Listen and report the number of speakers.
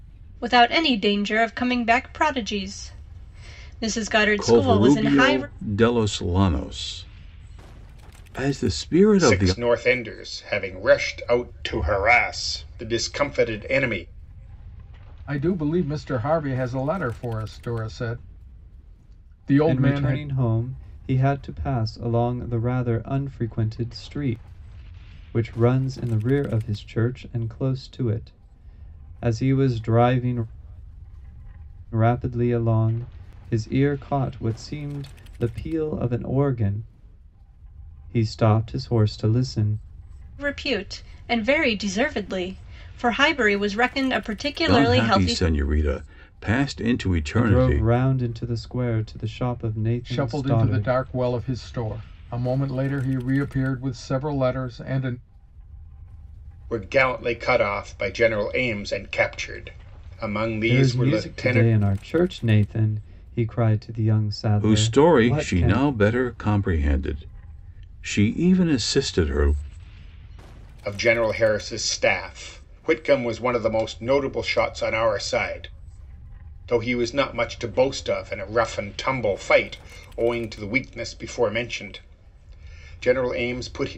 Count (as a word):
five